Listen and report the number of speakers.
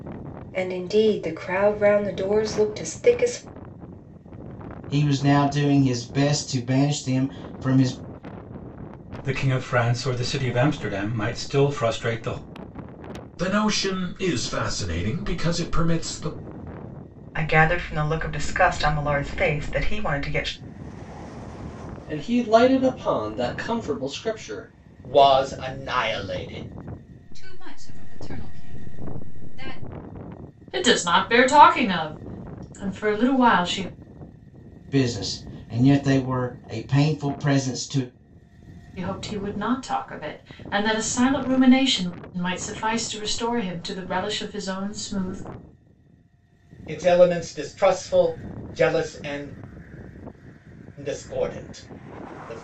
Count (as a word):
nine